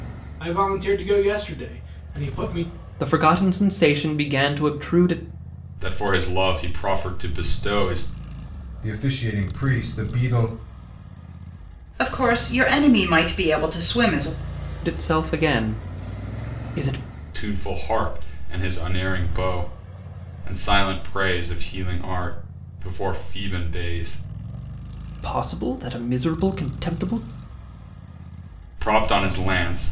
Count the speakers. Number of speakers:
5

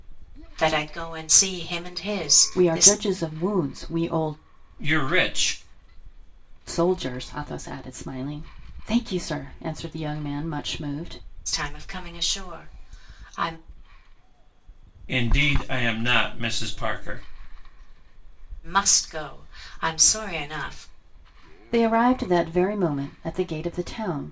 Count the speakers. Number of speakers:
3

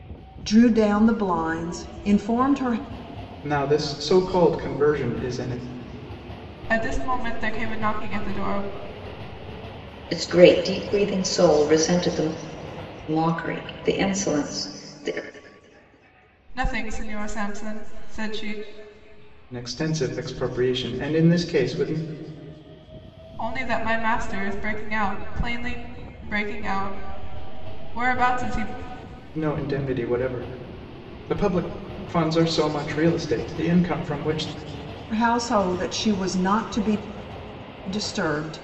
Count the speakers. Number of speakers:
4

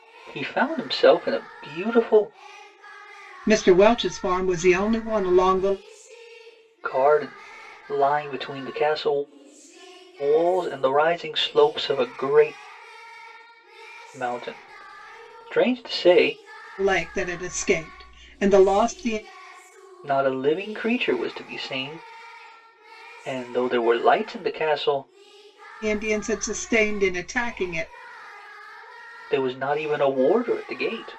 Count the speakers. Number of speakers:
2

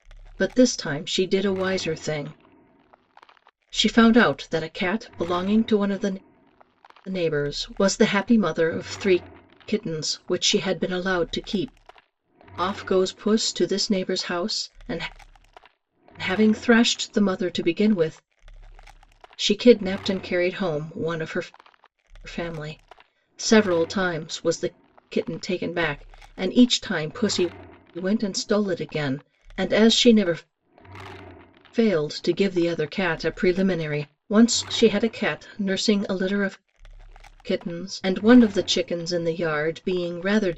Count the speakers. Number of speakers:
1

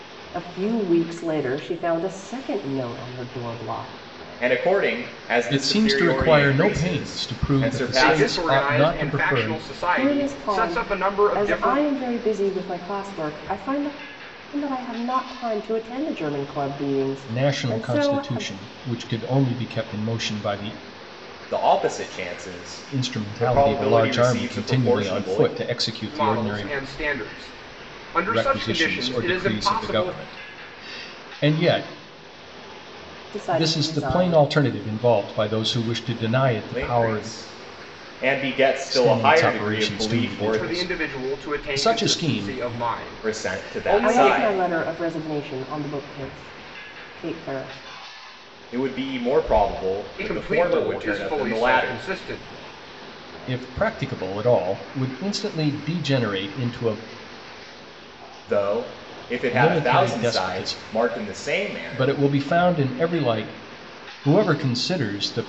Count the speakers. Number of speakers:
4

